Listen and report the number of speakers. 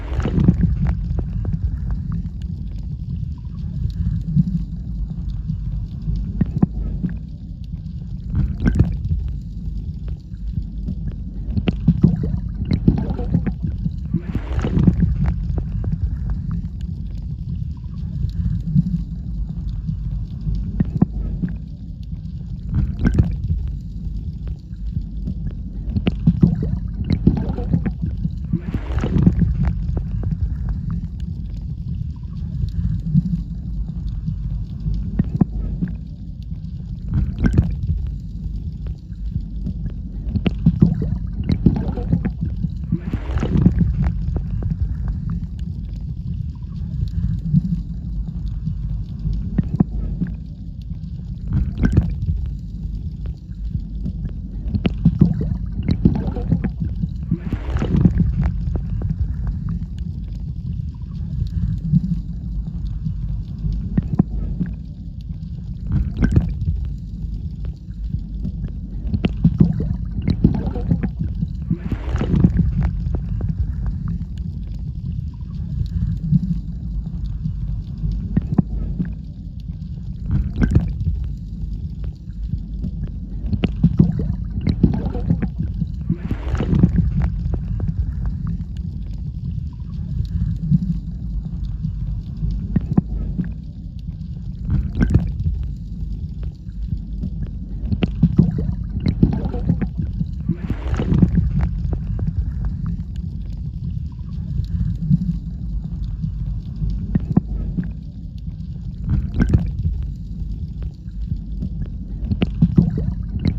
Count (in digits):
0